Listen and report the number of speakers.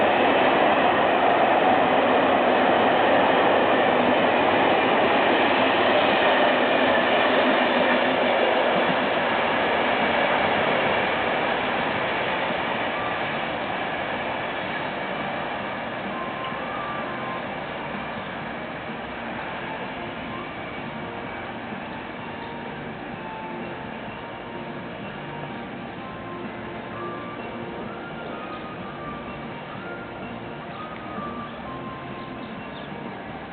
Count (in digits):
0